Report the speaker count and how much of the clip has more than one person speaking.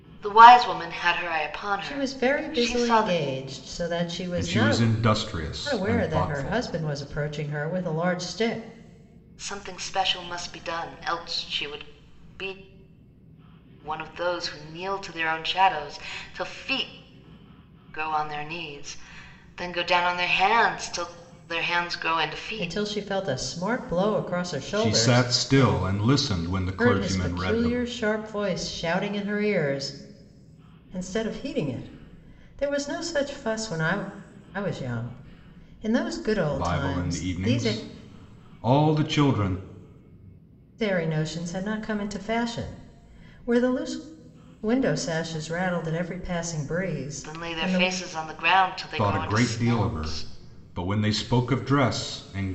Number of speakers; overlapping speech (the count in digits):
3, about 17%